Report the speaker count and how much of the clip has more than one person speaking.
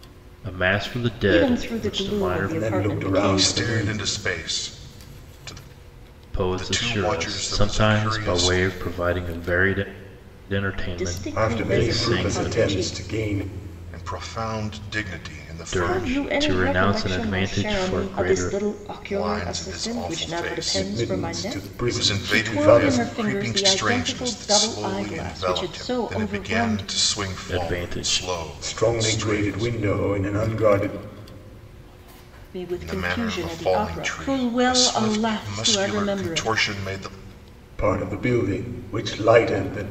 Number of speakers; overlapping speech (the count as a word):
four, about 60%